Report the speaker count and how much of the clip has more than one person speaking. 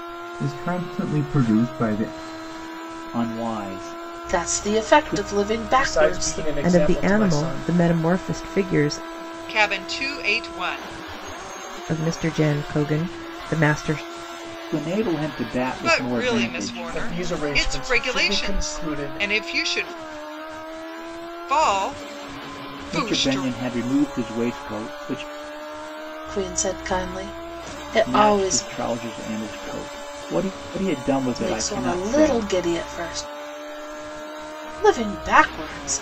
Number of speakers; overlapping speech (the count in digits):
6, about 24%